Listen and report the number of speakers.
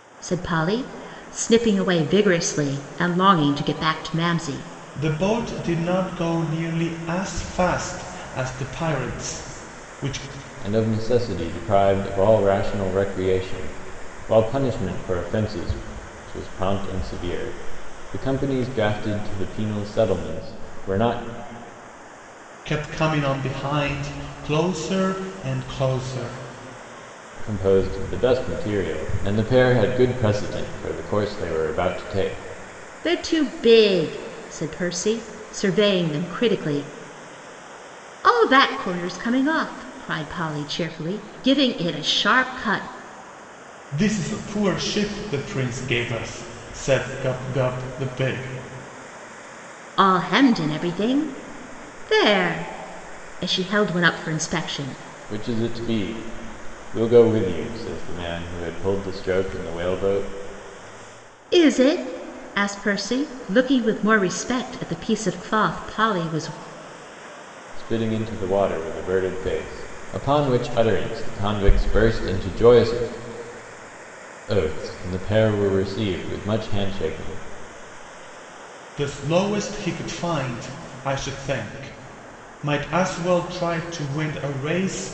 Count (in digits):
3